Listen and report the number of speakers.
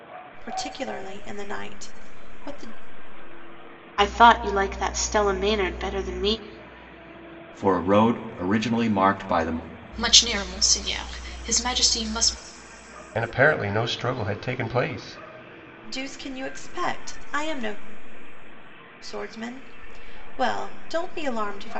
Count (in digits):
5